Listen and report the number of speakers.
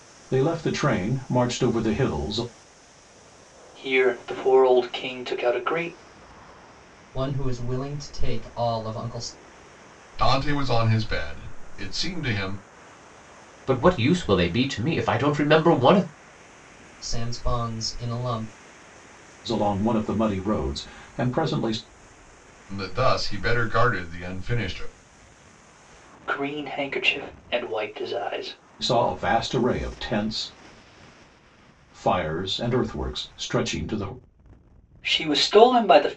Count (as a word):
five